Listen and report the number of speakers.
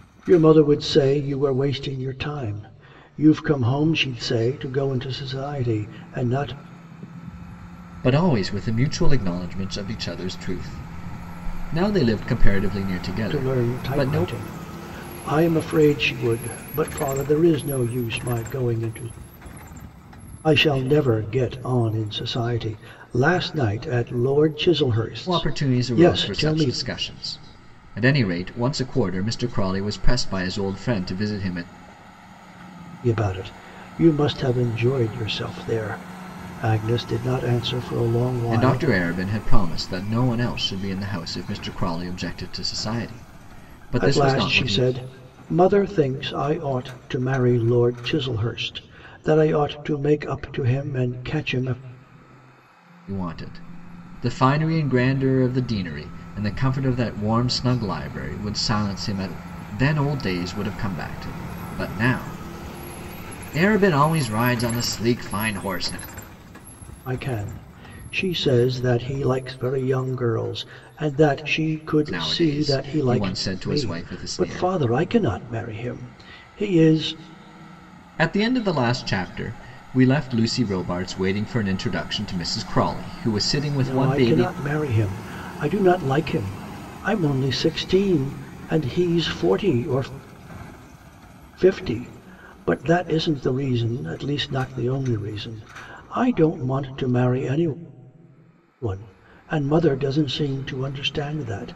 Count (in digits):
2